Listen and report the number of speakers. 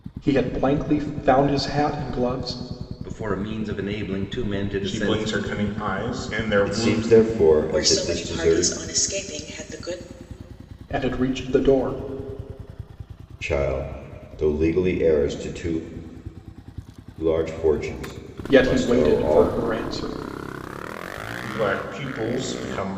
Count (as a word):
five